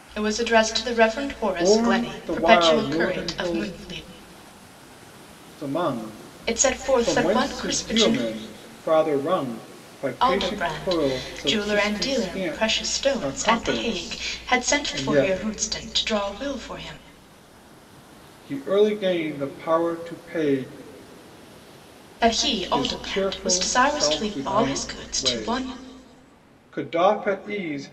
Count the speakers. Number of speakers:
2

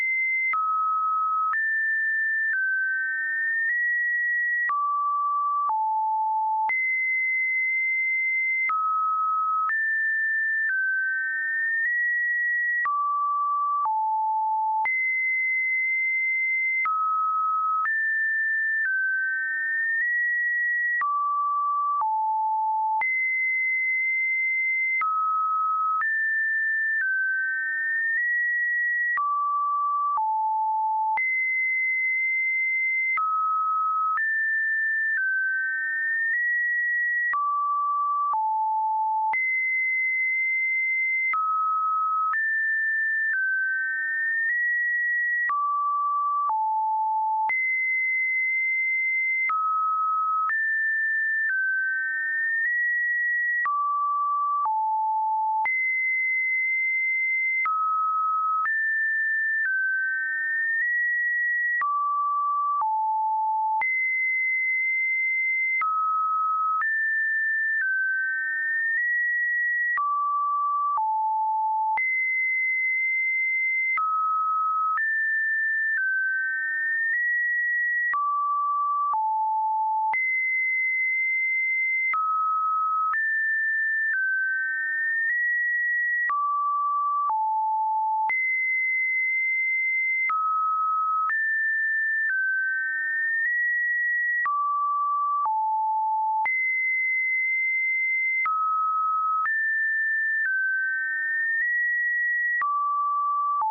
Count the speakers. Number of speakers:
0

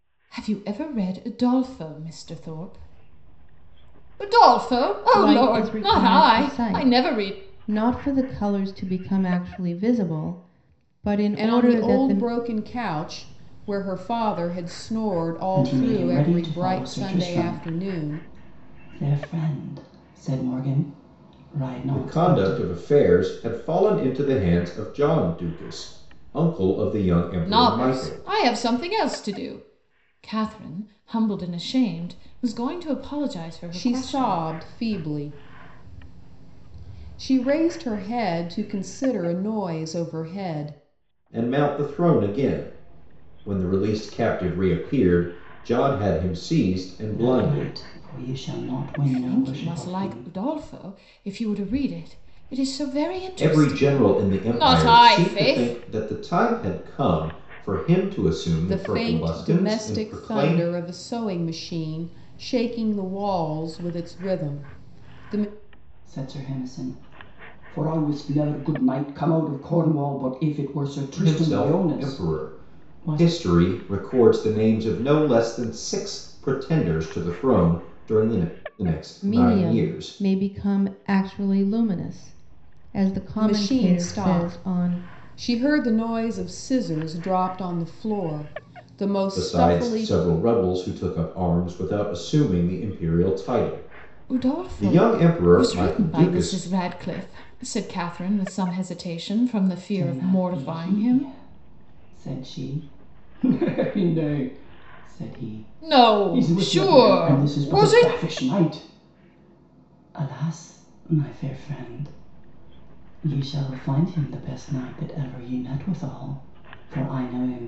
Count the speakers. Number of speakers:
5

